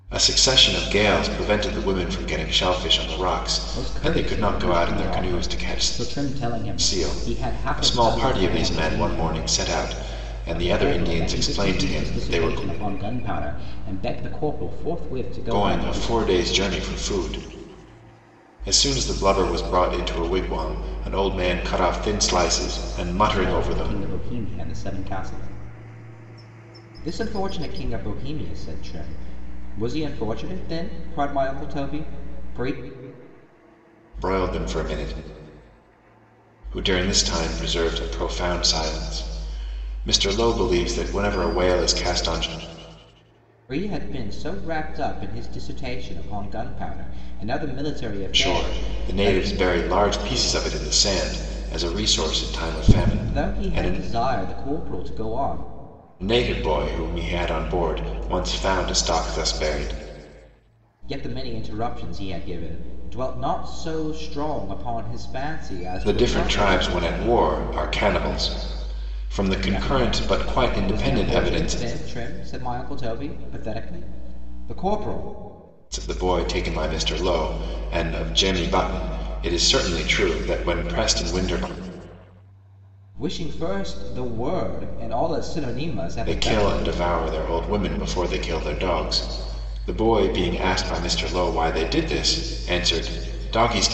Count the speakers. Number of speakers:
two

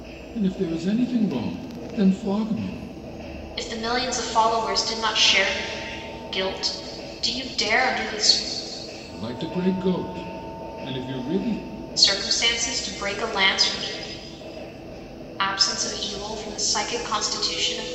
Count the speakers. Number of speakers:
two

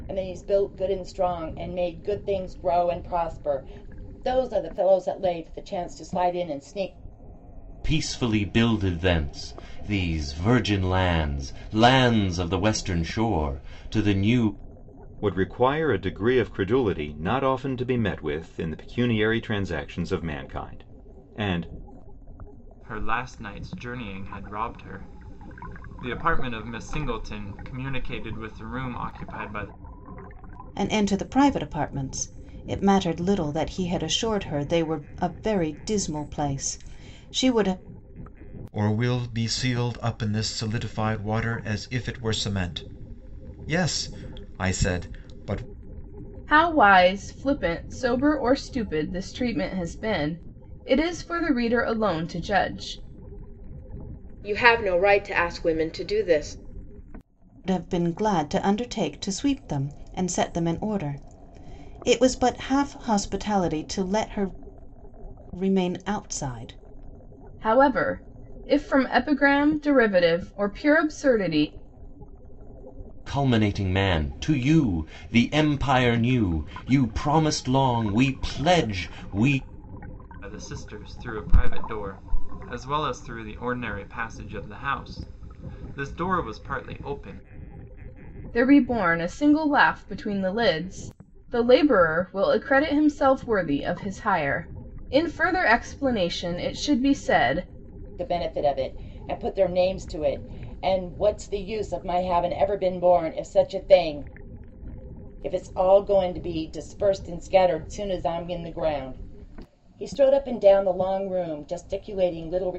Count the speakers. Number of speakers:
eight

